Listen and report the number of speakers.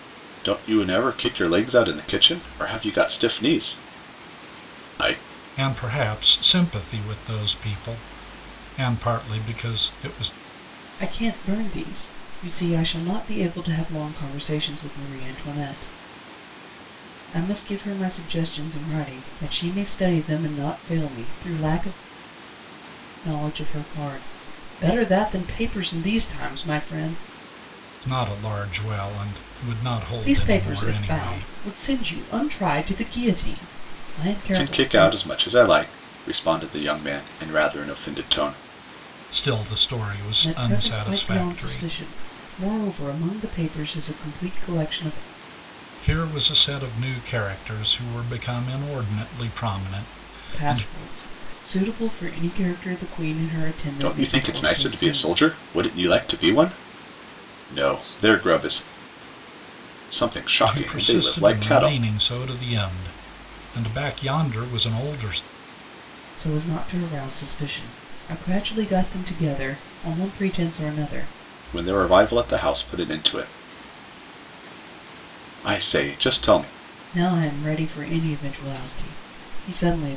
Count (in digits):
3